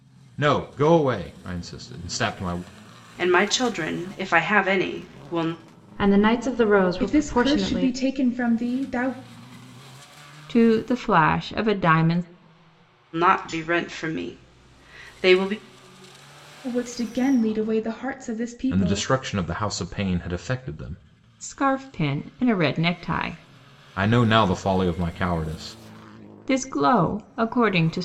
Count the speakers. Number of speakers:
5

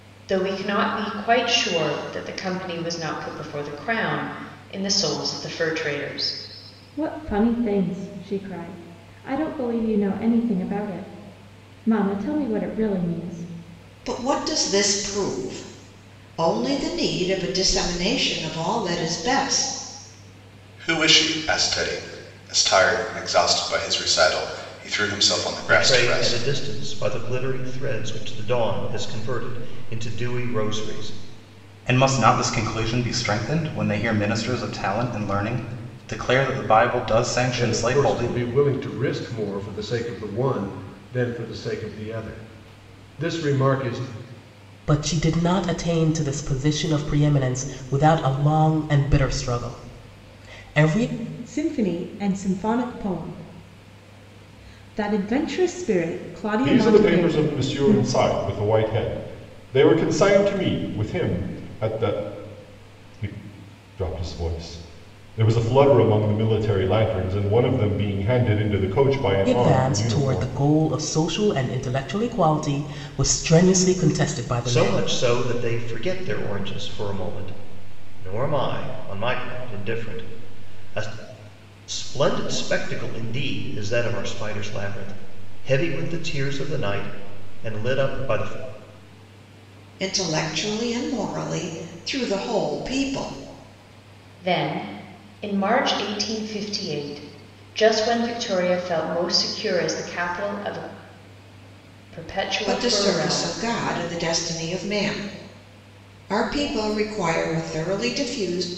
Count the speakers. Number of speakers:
10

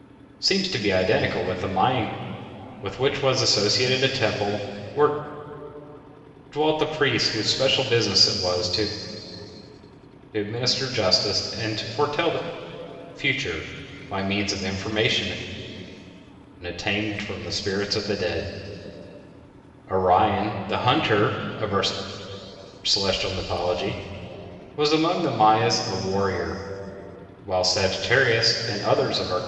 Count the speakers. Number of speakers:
1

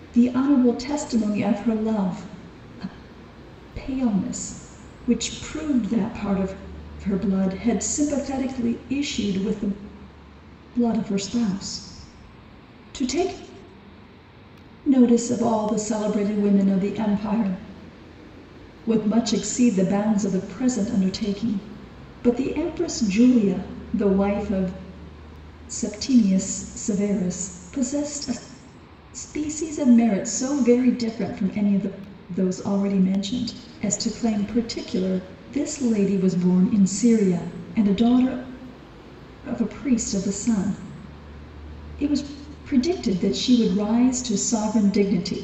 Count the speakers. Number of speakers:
1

